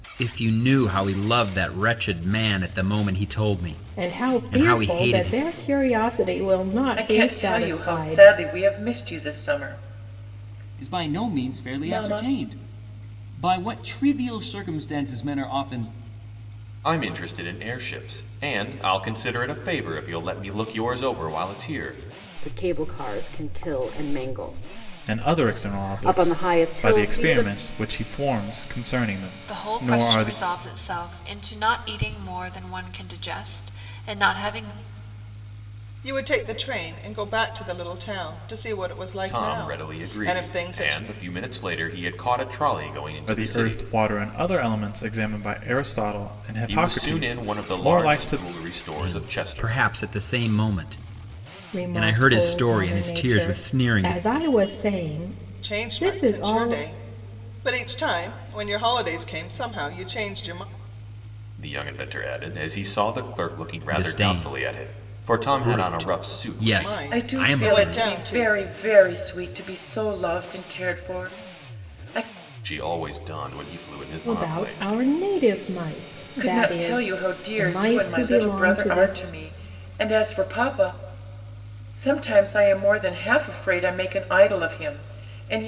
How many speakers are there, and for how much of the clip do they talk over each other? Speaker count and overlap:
nine, about 29%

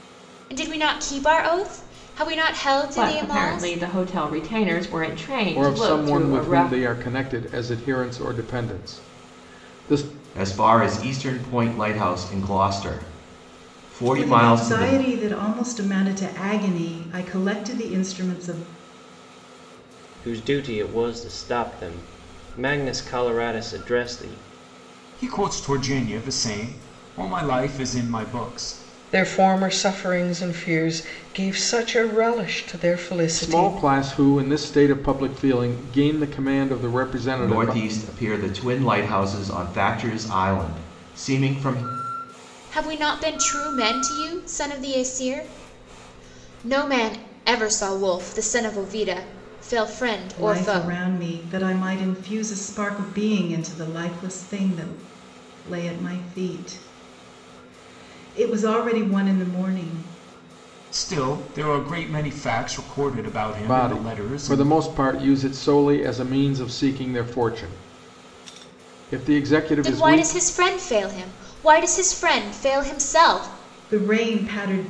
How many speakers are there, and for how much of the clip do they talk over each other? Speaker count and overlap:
eight, about 8%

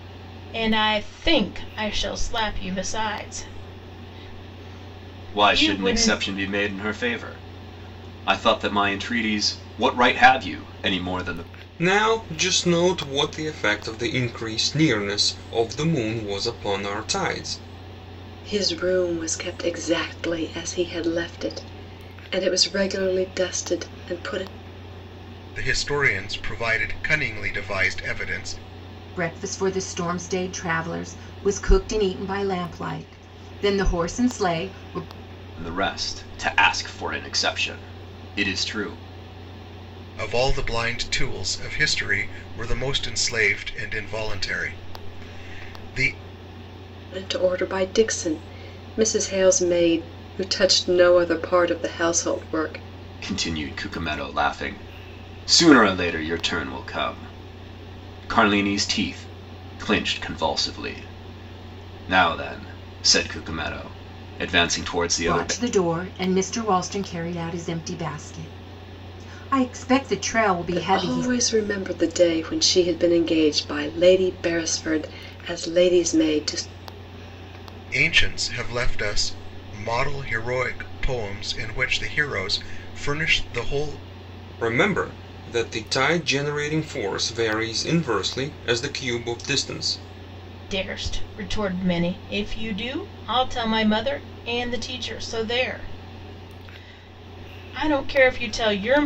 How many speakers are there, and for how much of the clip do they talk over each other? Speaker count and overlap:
six, about 2%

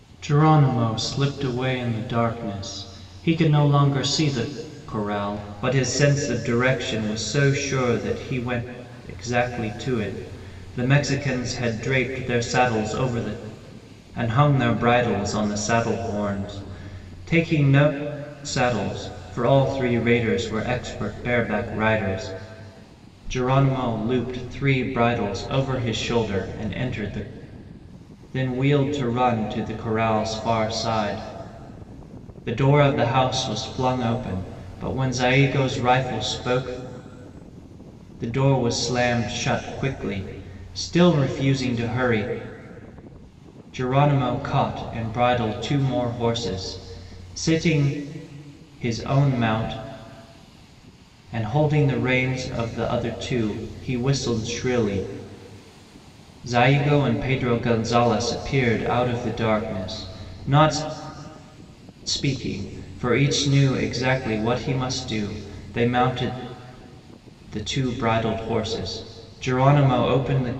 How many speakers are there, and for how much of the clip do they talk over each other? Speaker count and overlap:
one, no overlap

